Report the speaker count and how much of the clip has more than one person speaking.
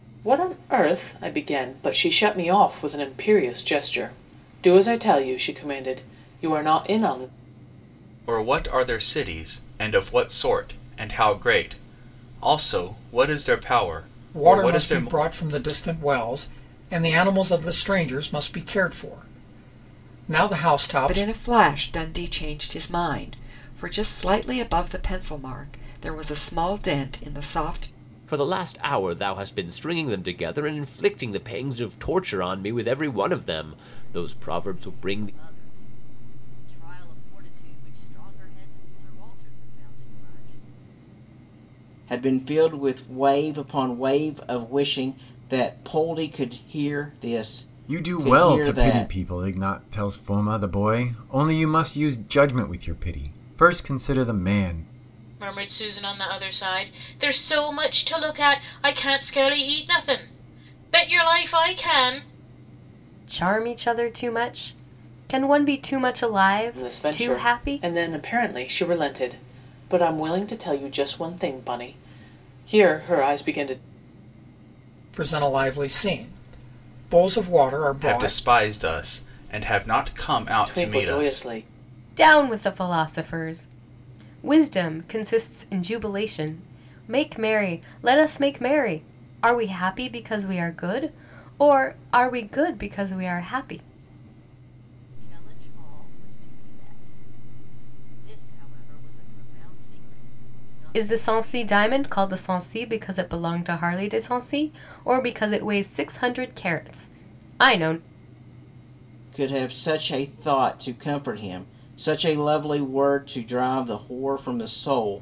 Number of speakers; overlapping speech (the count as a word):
ten, about 7%